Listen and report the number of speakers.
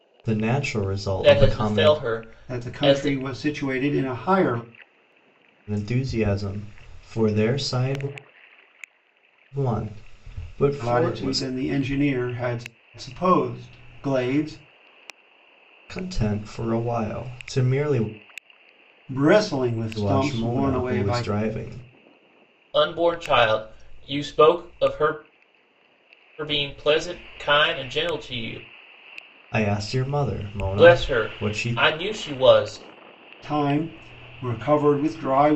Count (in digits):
3